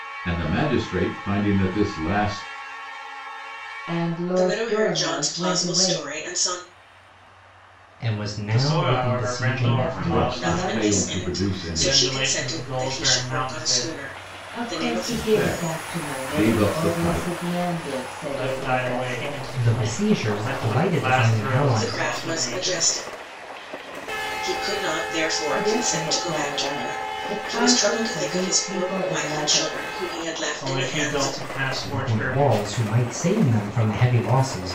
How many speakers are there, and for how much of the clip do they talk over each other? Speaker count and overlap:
five, about 57%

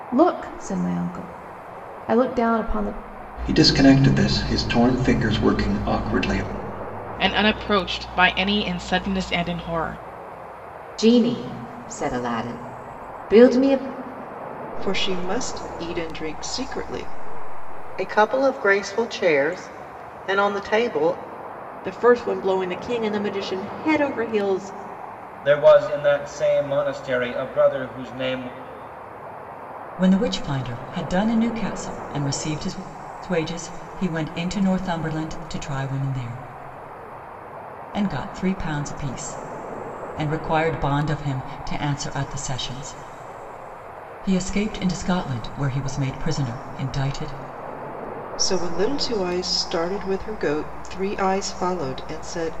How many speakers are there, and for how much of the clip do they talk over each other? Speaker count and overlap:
nine, no overlap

